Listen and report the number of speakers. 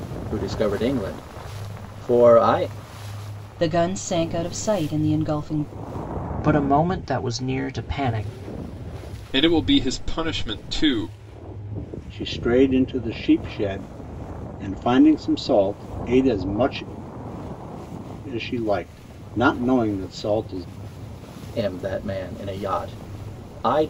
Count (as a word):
five